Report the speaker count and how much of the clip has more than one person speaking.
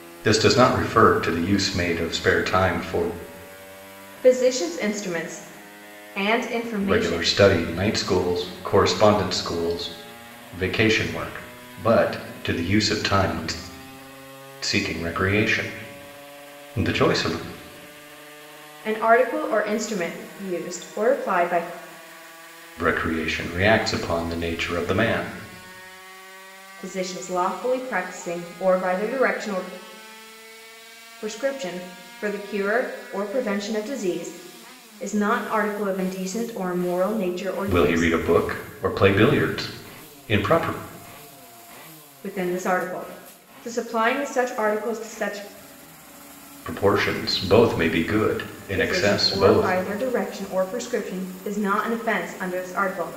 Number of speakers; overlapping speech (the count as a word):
two, about 4%